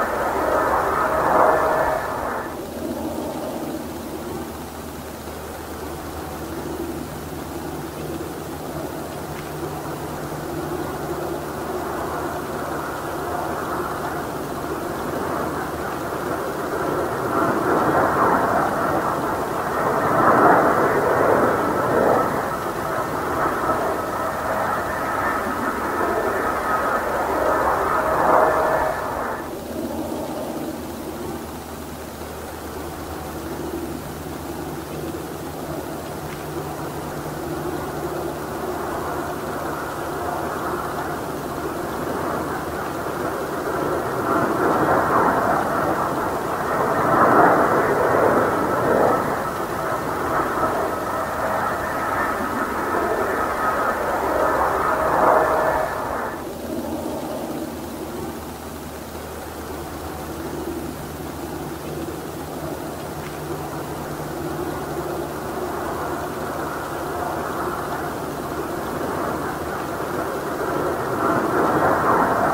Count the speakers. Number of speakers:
0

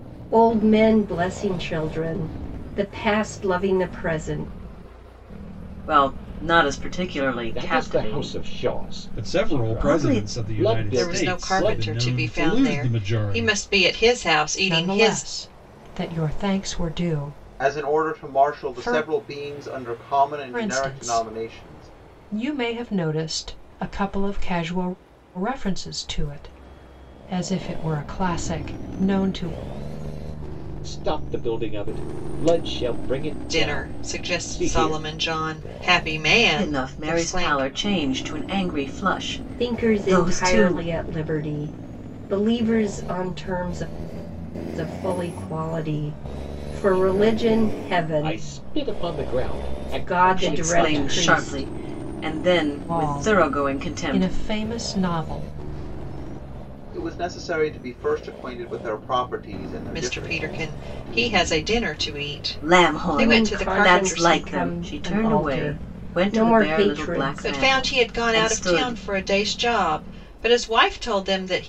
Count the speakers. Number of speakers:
7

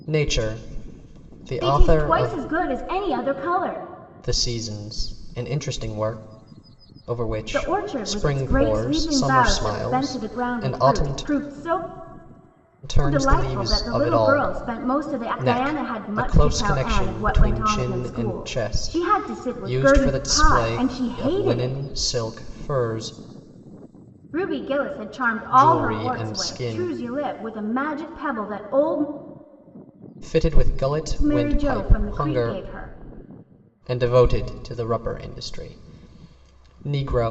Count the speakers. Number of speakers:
2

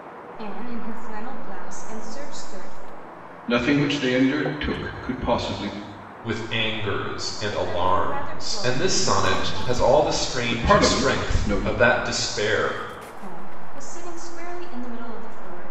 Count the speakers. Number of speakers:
3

